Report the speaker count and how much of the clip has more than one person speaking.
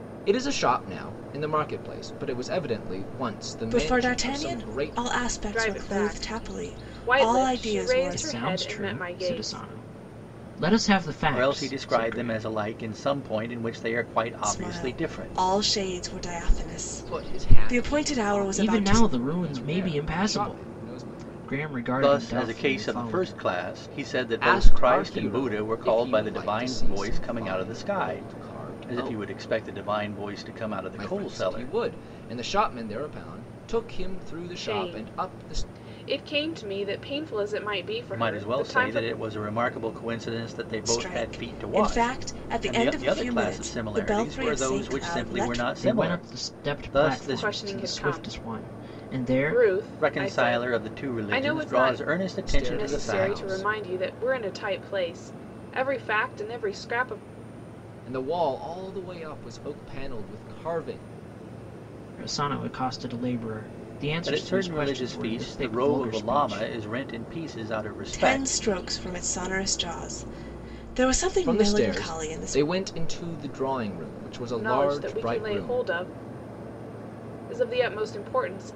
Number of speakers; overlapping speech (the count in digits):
5, about 50%